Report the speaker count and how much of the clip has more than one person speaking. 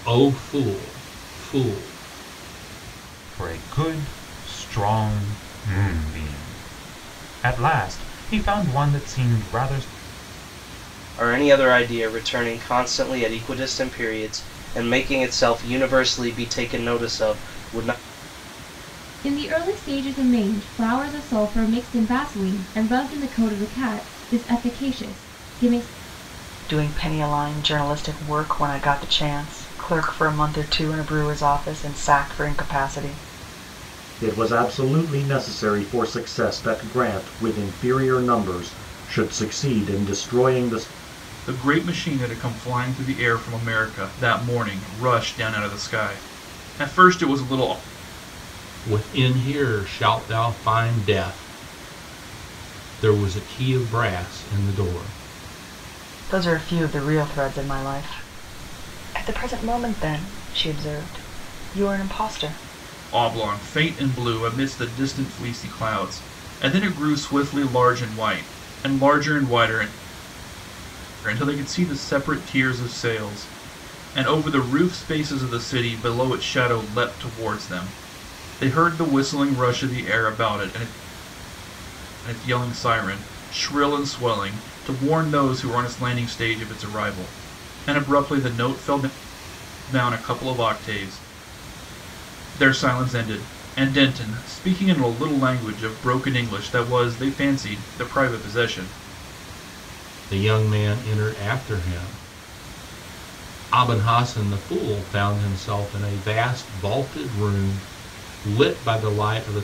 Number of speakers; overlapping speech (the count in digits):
7, no overlap